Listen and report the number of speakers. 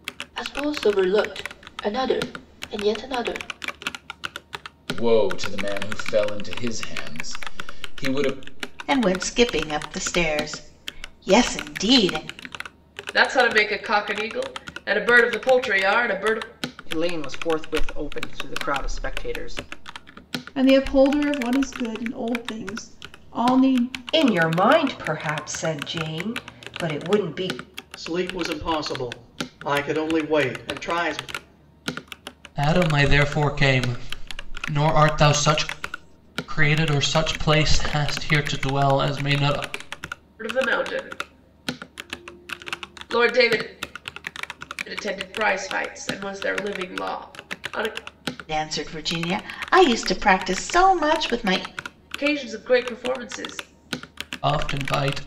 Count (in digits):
9